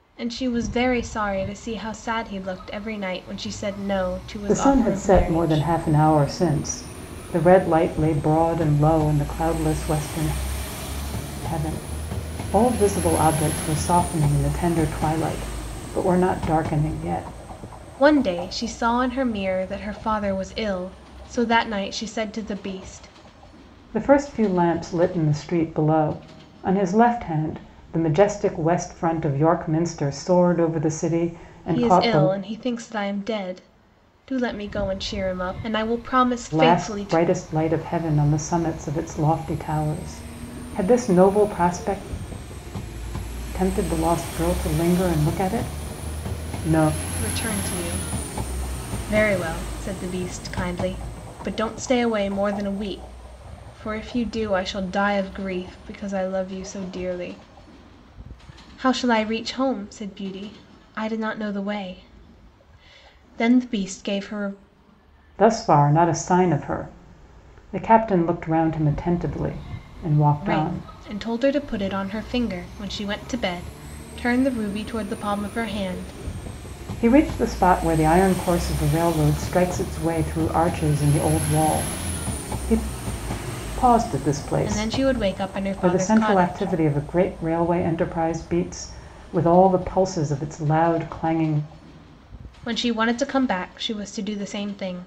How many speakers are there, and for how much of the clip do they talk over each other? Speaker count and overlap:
two, about 5%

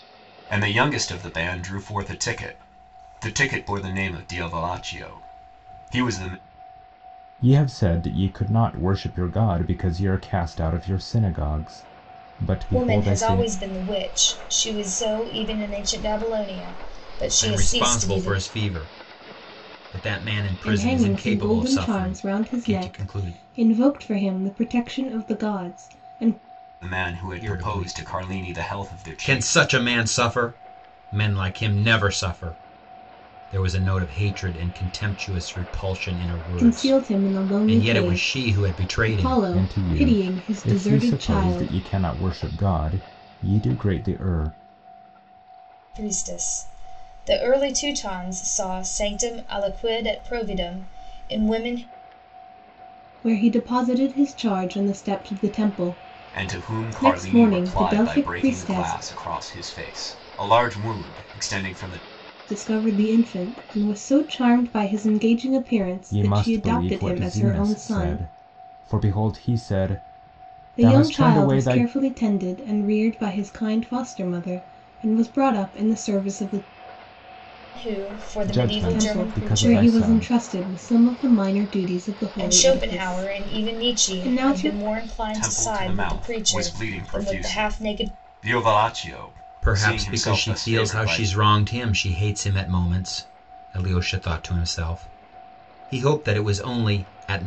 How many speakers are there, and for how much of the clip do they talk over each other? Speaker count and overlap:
five, about 28%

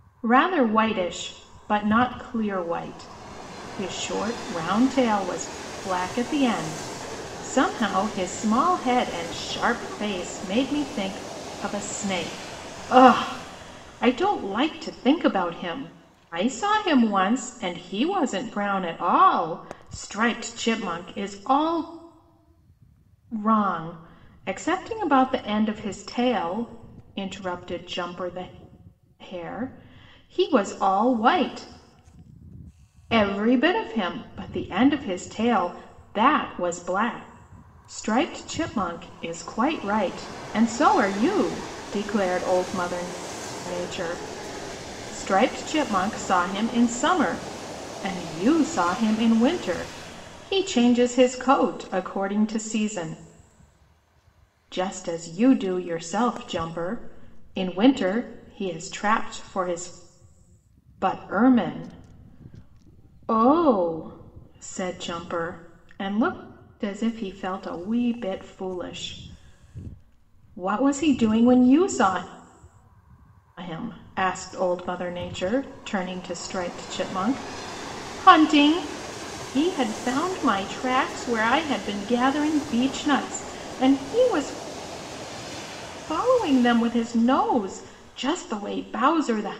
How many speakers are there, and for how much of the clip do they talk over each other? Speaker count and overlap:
one, no overlap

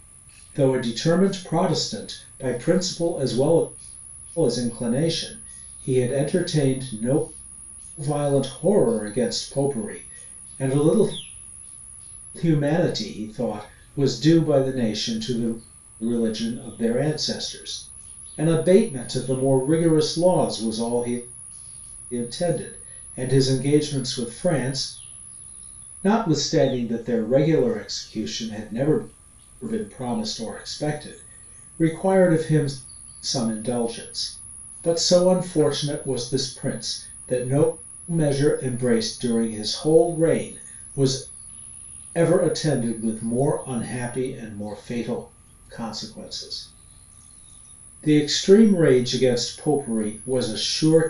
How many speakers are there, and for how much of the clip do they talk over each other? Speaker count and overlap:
one, no overlap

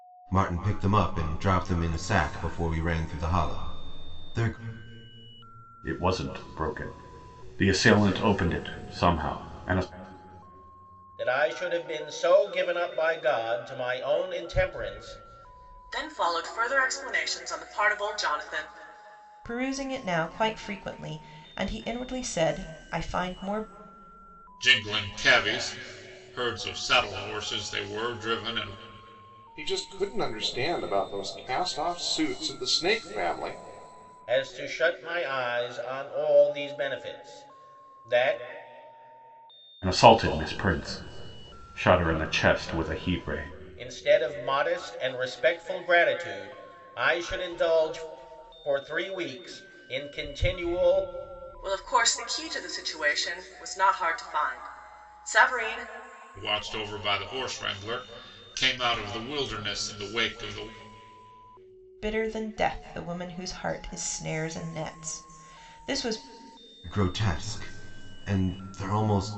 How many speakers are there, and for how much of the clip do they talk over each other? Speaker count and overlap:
seven, no overlap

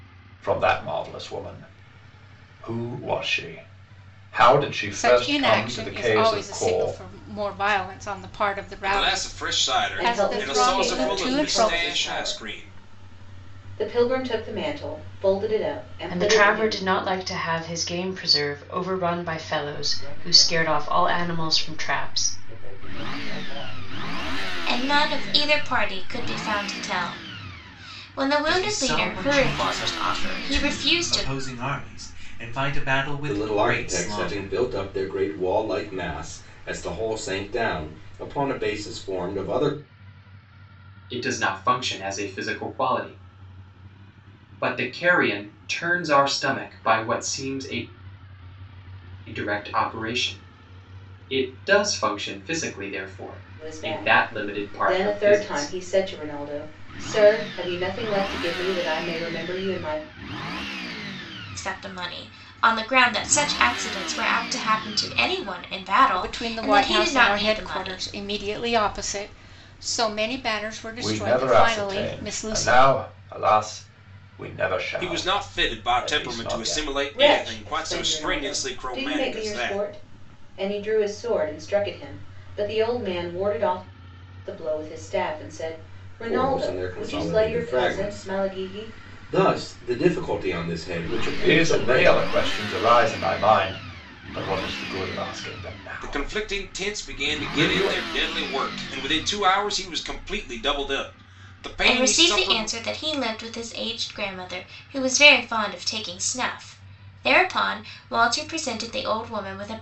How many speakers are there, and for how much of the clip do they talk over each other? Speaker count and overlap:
ten, about 30%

